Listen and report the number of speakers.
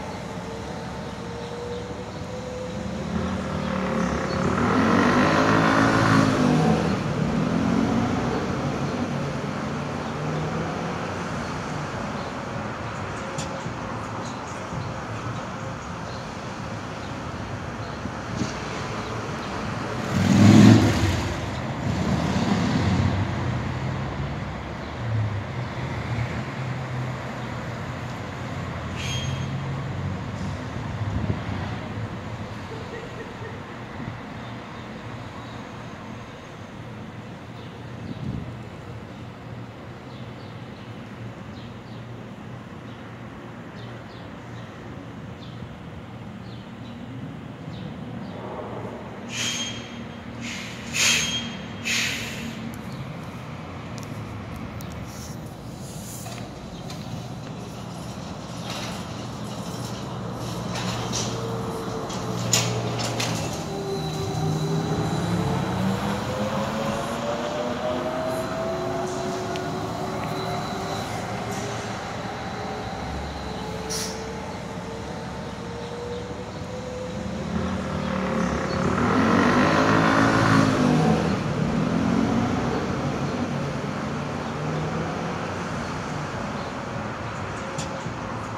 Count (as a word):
zero